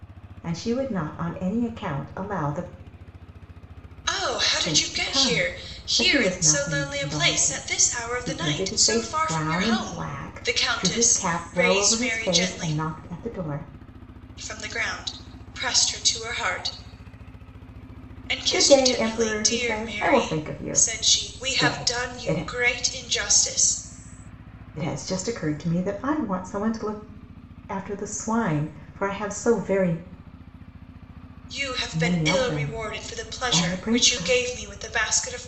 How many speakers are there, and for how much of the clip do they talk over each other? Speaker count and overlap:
2, about 40%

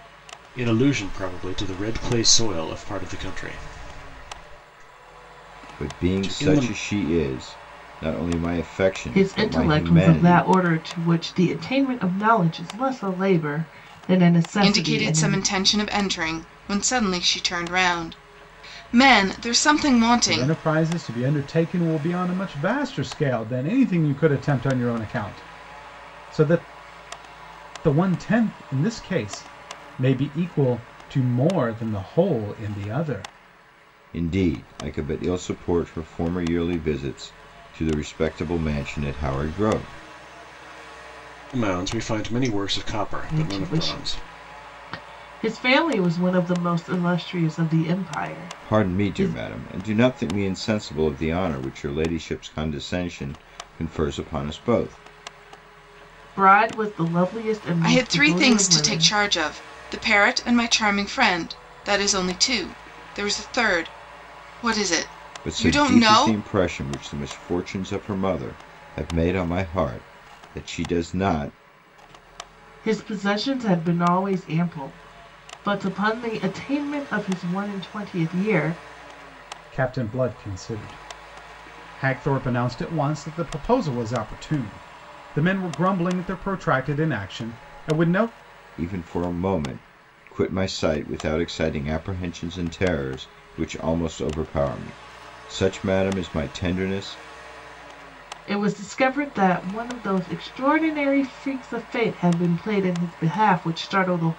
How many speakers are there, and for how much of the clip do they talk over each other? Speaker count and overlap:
5, about 7%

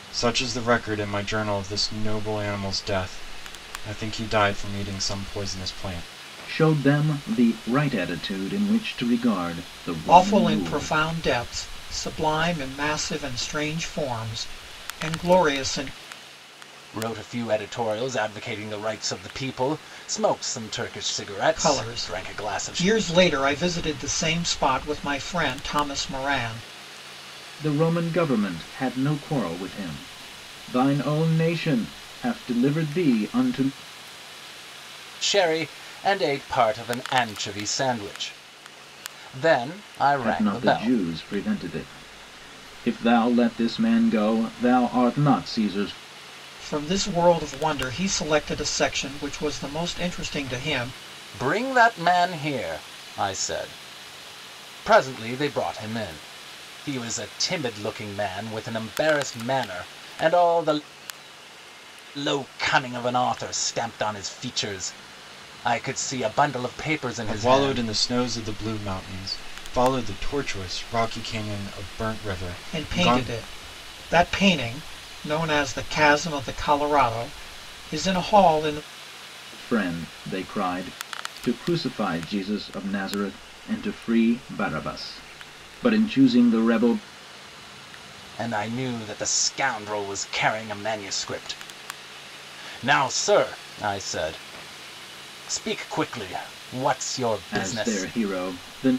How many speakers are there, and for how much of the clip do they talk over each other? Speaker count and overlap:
4, about 5%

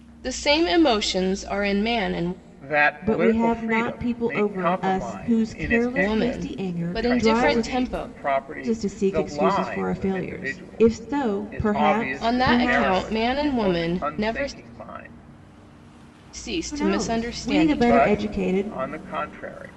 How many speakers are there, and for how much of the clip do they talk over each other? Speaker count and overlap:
3, about 66%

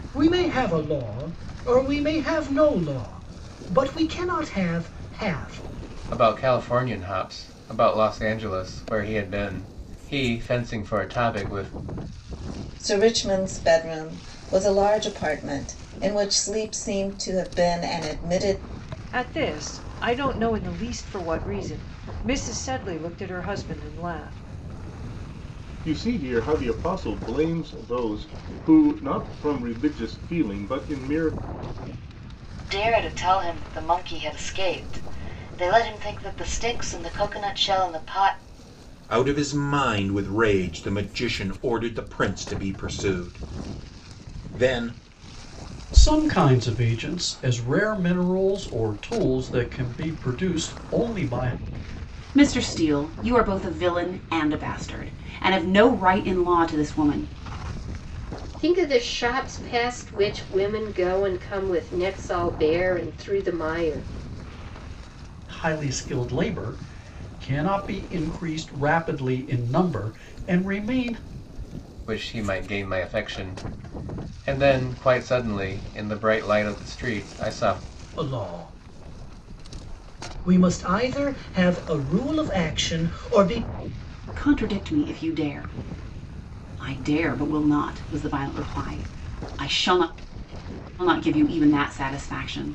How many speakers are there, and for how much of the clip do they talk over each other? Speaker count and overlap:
10, no overlap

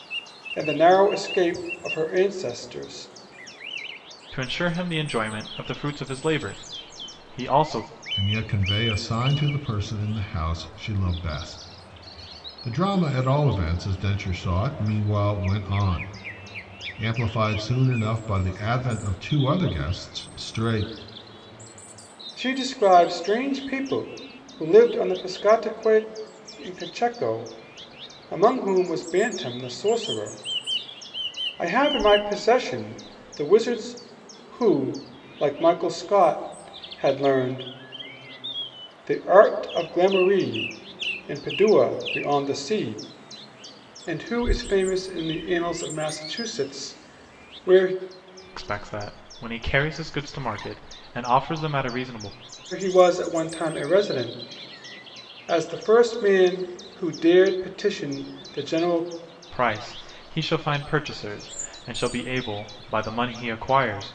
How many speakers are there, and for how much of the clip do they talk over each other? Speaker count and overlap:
3, no overlap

